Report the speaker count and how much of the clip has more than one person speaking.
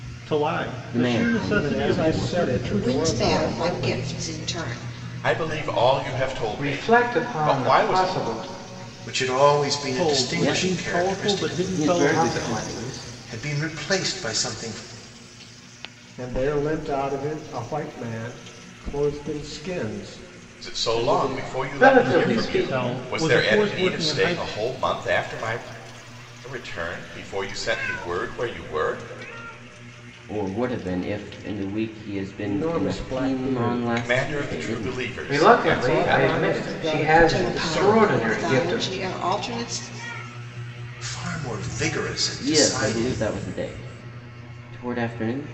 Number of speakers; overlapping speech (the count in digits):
7, about 41%